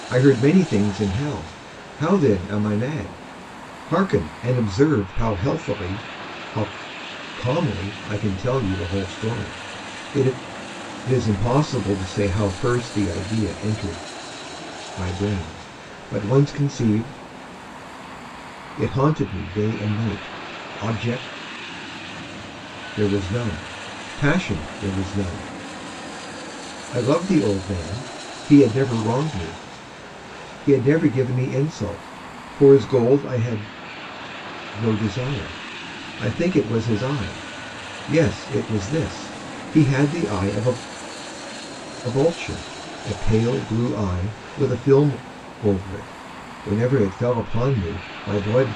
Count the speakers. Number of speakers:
1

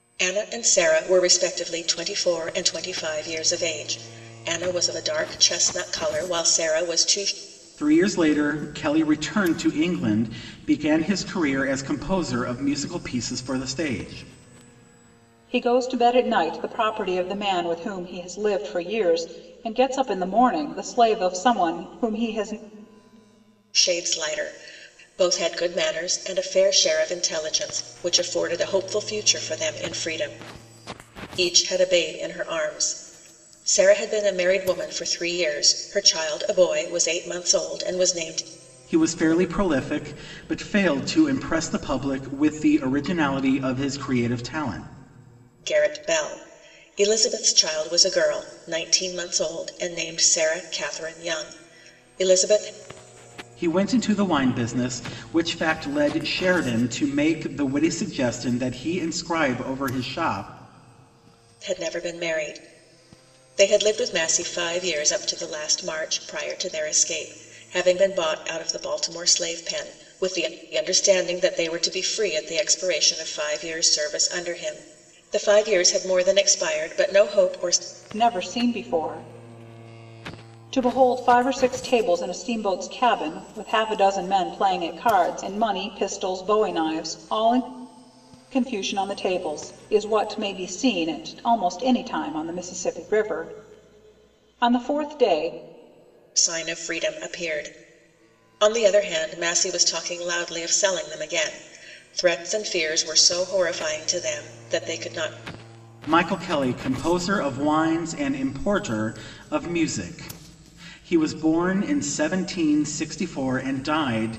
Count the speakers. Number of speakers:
3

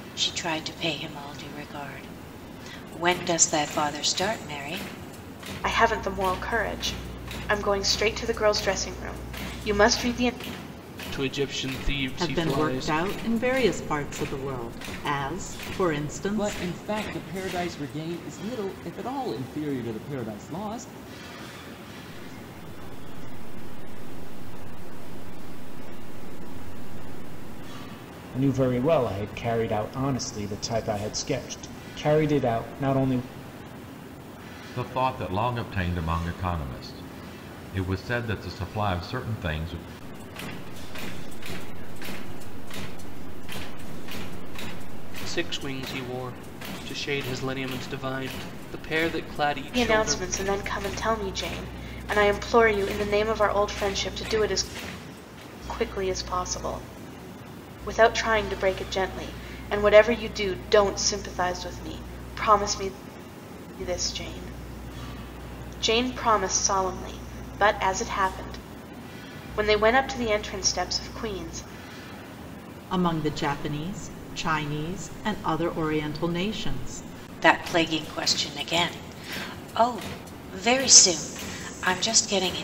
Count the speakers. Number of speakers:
8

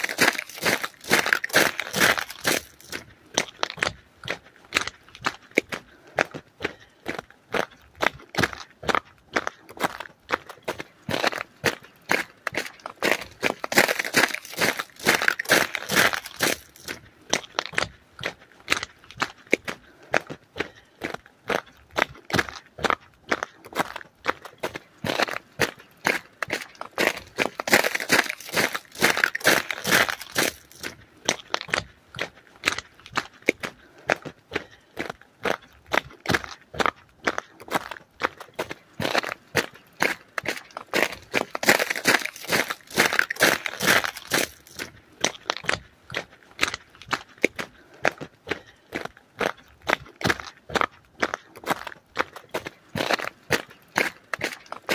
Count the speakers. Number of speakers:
0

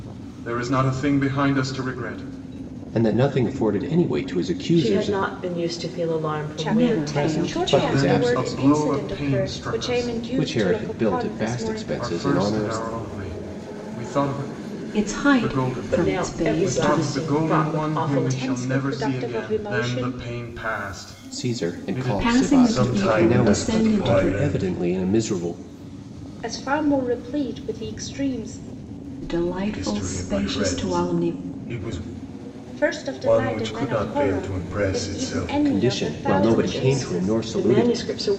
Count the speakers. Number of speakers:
5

